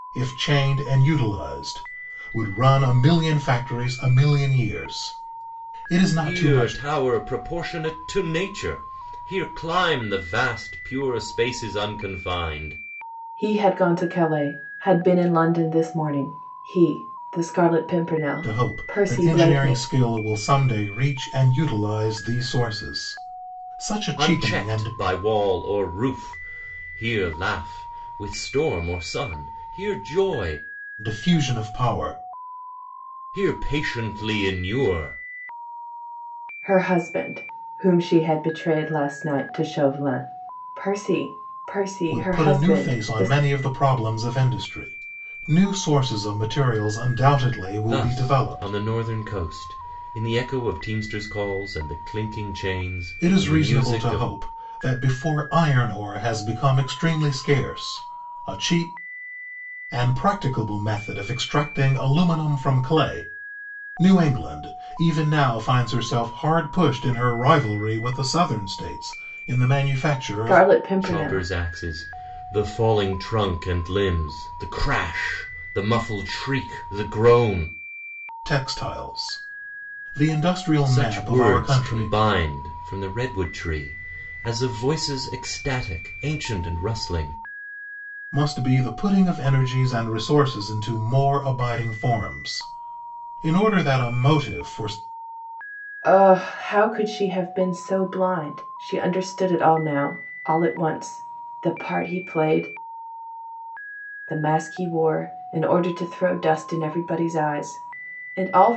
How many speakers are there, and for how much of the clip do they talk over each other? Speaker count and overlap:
three, about 8%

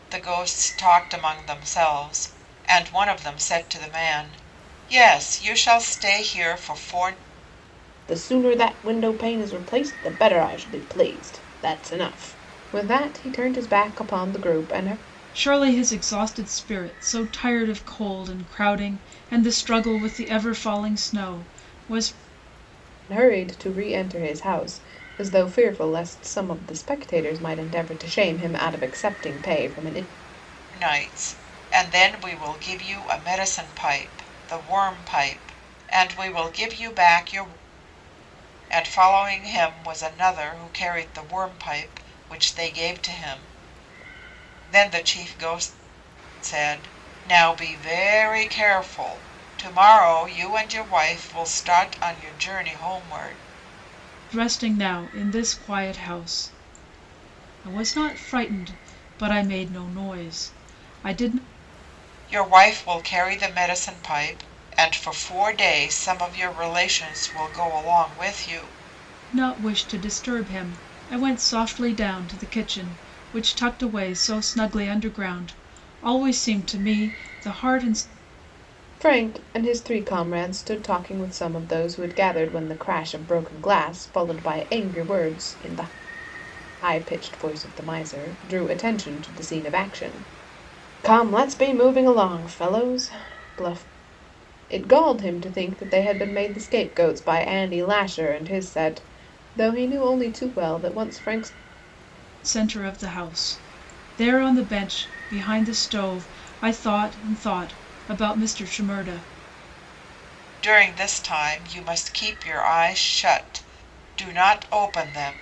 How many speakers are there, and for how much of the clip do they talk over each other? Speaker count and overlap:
three, no overlap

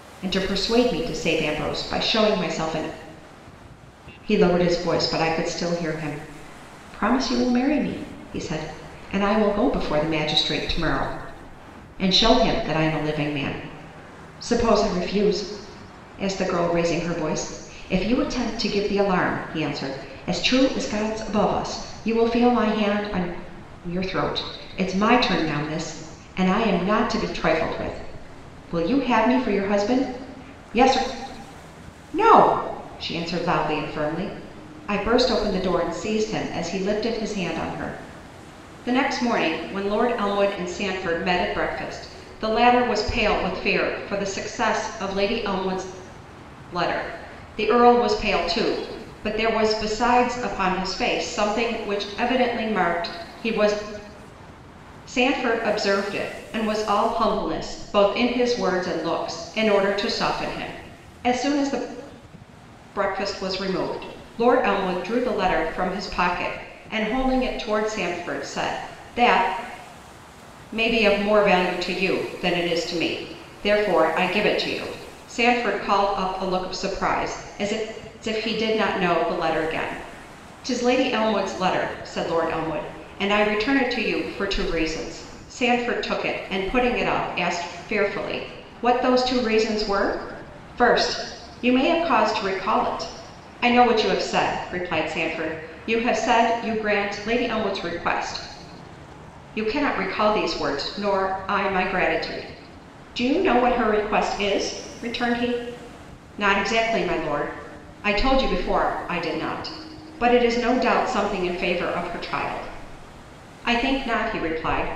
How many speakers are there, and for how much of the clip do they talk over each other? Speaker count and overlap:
one, no overlap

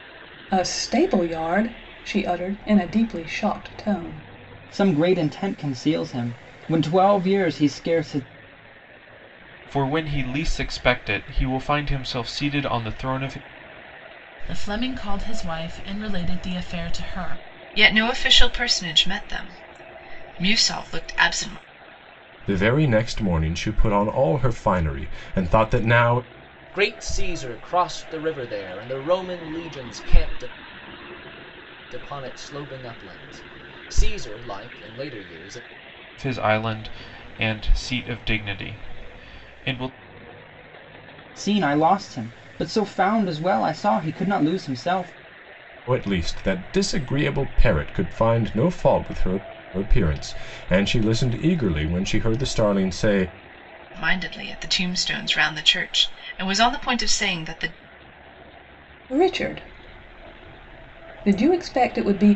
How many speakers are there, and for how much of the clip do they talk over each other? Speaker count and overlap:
seven, no overlap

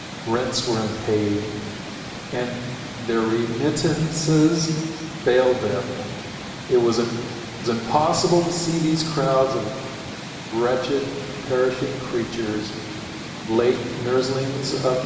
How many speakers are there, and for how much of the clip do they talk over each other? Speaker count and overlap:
one, no overlap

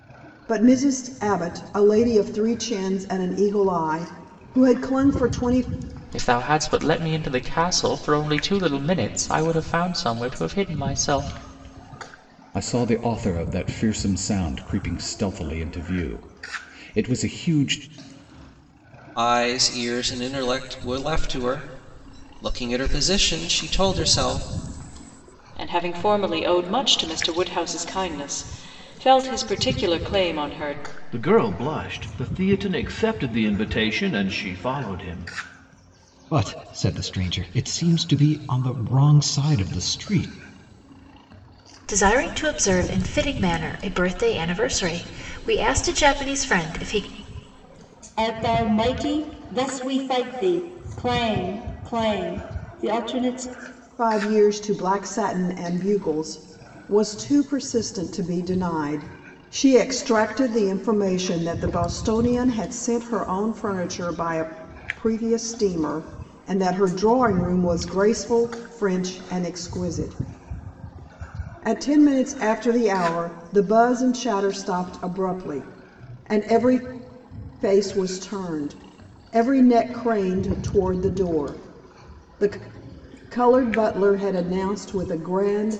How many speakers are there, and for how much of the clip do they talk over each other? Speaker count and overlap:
nine, no overlap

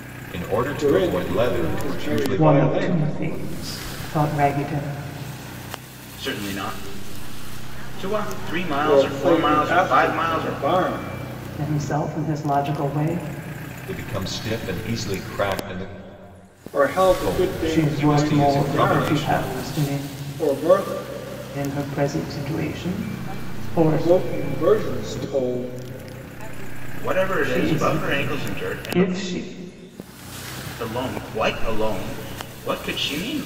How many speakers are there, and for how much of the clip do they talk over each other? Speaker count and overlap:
five, about 41%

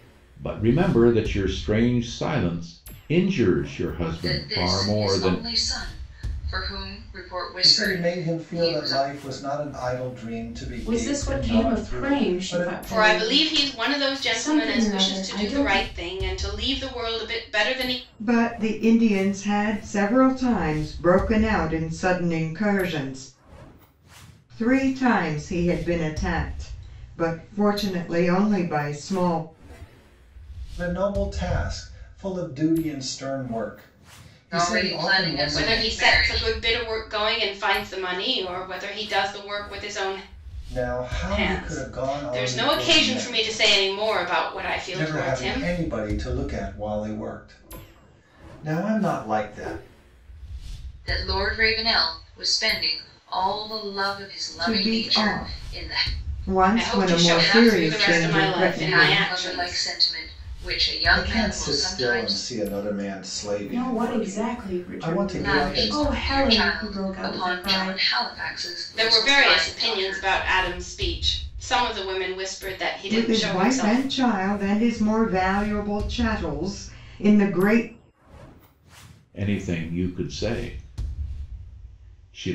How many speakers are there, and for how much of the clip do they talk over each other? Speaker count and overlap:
six, about 31%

